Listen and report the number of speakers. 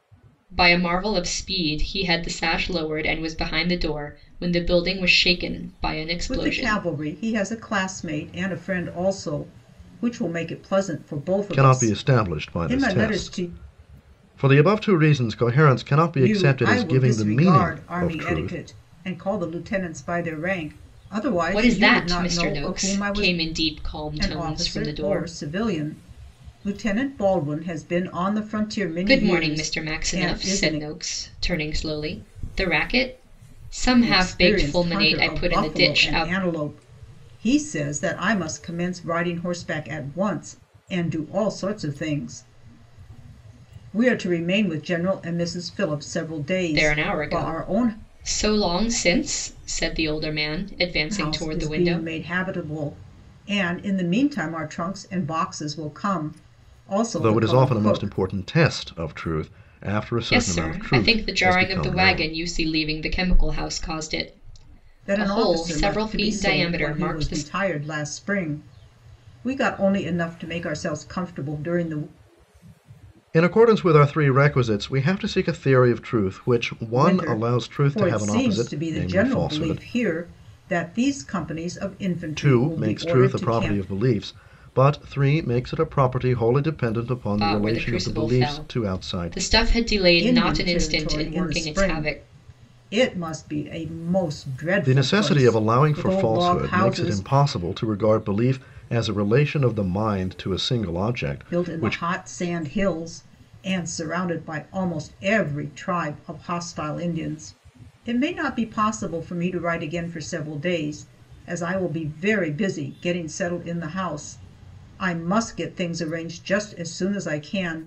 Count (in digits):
3